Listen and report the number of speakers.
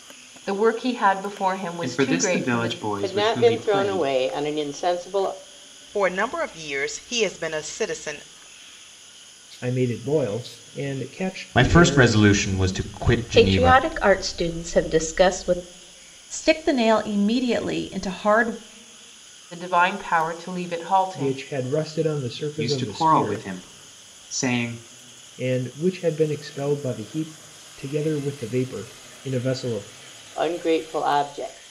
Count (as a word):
eight